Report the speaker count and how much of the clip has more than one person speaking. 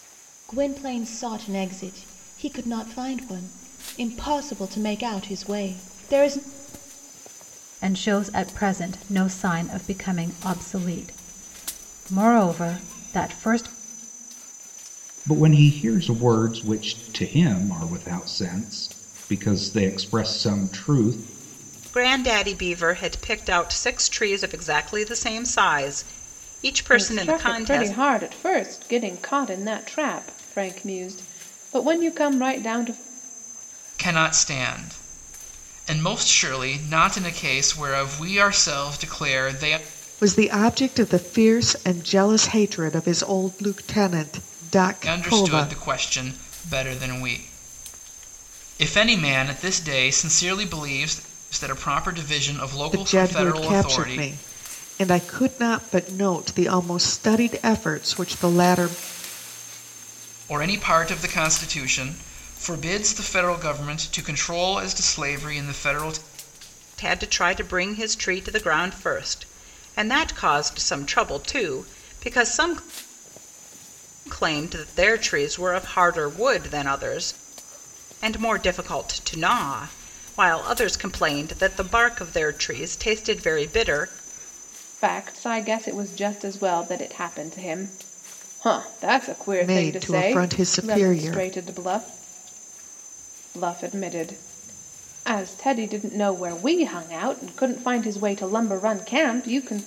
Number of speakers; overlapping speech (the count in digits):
7, about 5%